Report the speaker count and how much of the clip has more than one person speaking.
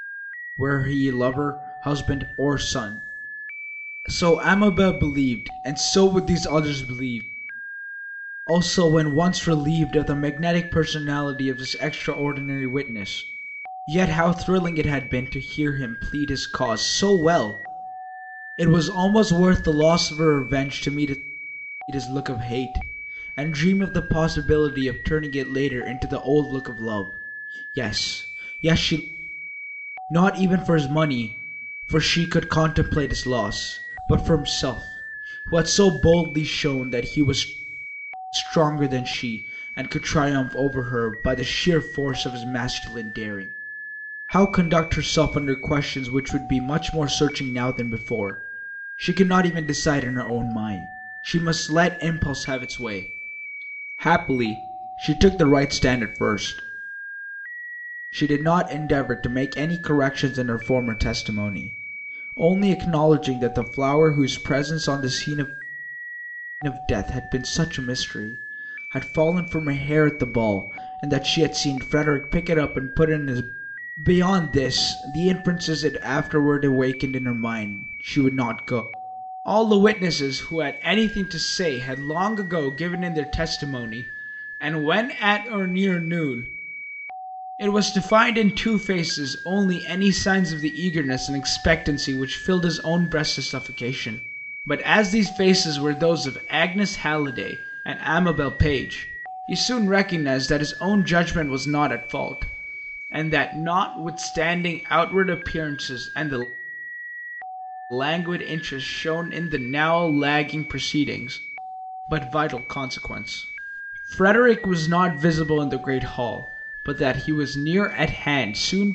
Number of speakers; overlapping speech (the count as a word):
one, no overlap